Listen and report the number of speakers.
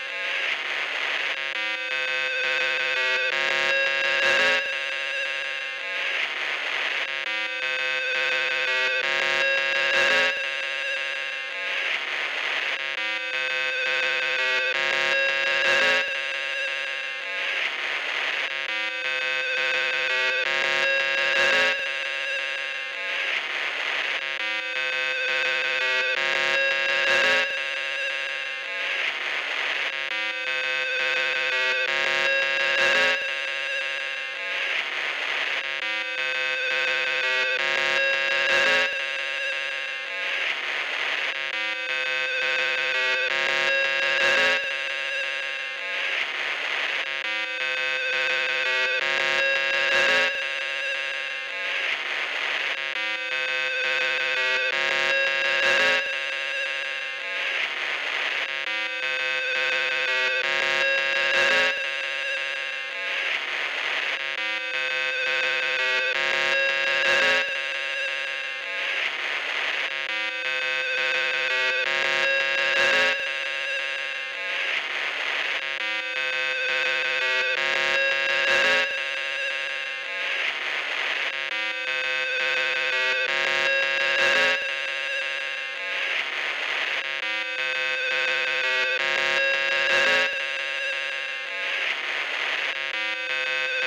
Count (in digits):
0